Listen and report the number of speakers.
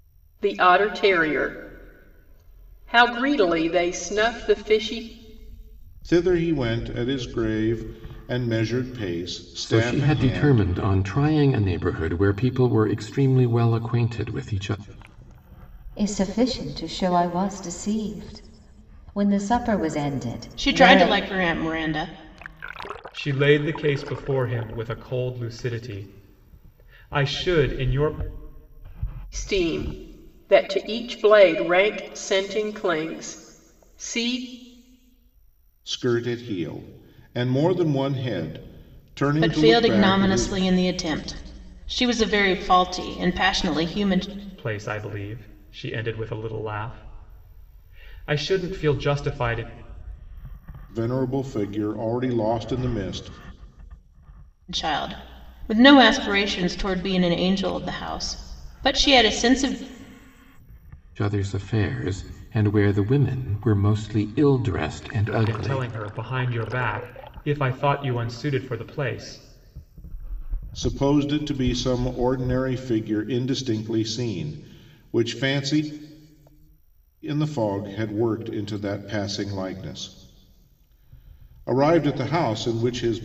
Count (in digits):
6